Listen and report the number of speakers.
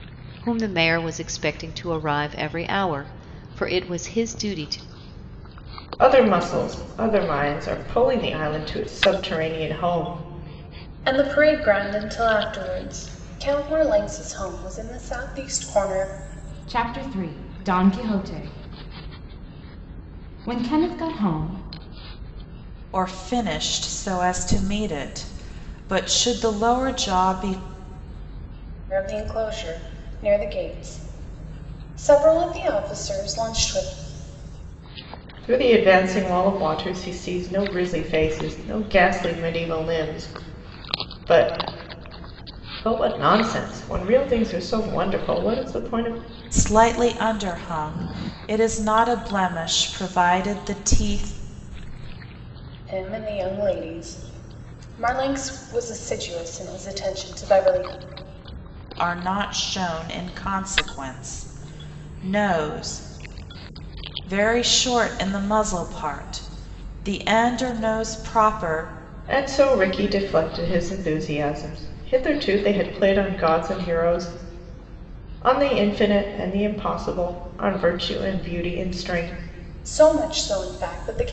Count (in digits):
5